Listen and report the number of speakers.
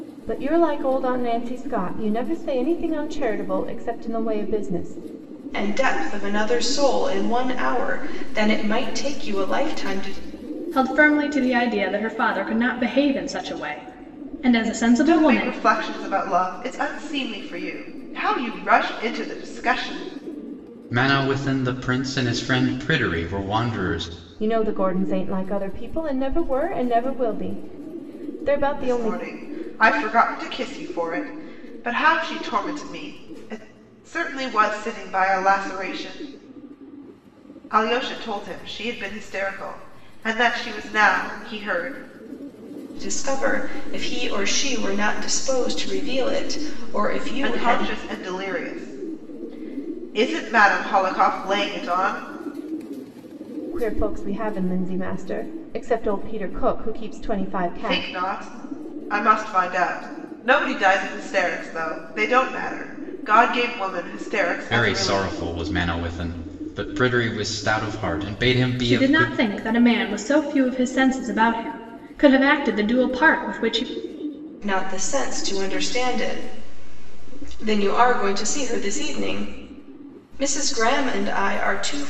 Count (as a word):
five